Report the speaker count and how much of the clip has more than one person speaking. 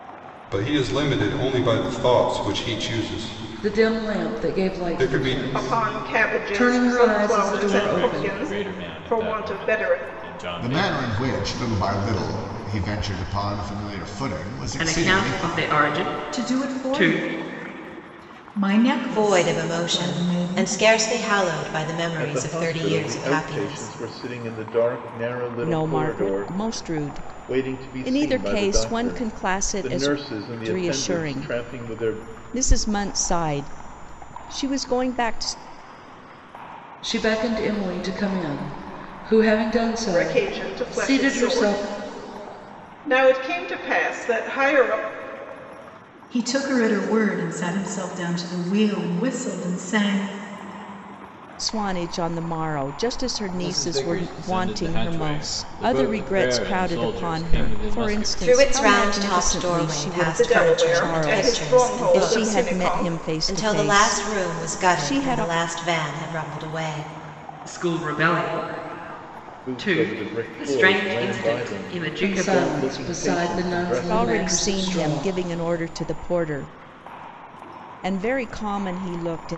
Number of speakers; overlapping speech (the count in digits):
10, about 47%